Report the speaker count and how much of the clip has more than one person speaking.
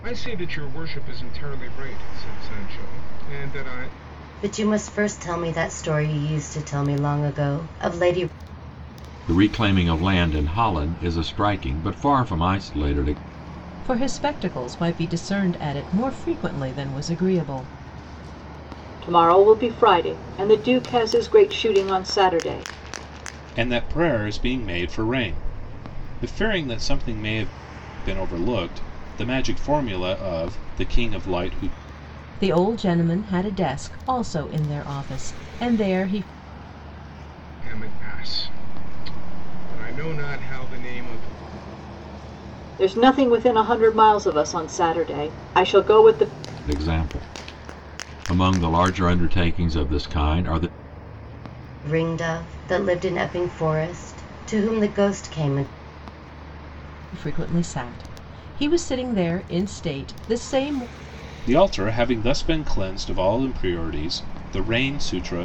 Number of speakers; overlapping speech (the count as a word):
six, no overlap